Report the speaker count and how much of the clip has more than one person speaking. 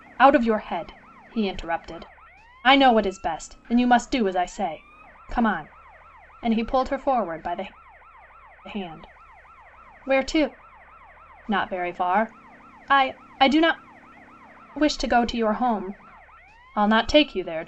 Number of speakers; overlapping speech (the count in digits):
1, no overlap